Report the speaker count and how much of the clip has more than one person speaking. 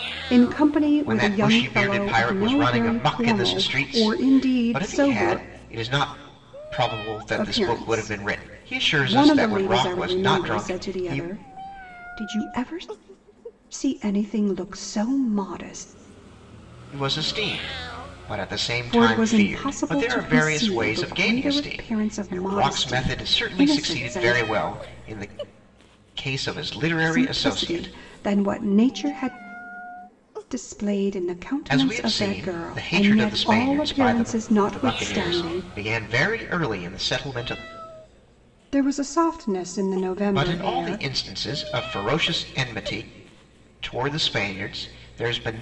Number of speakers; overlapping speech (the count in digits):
2, about 42%